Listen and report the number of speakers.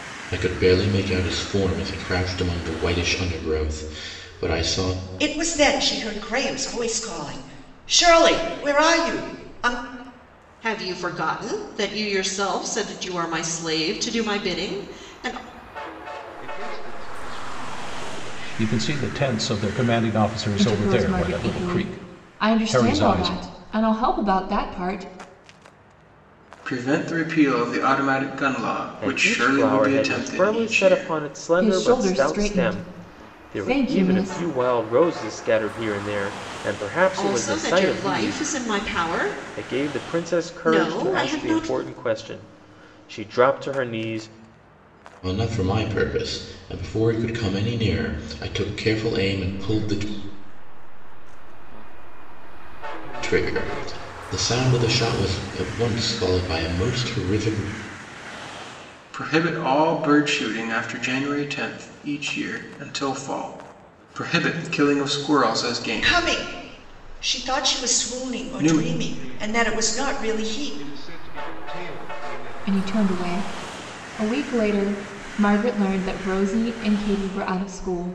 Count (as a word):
eight